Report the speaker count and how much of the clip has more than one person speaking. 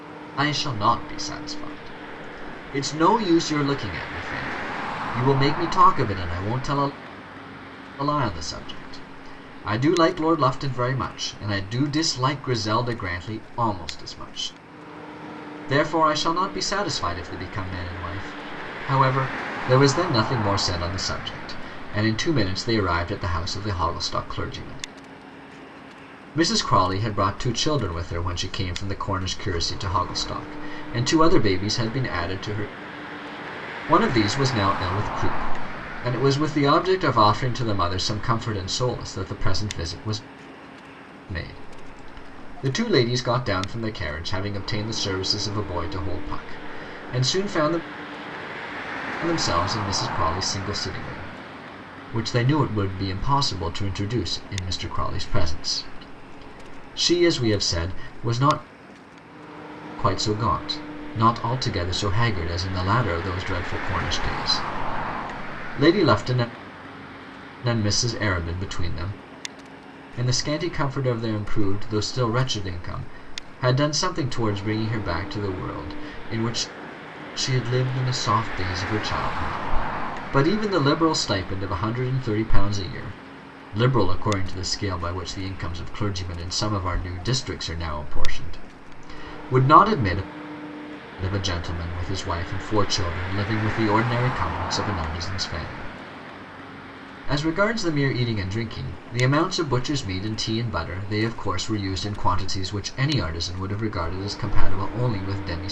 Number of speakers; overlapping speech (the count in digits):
1, no overlap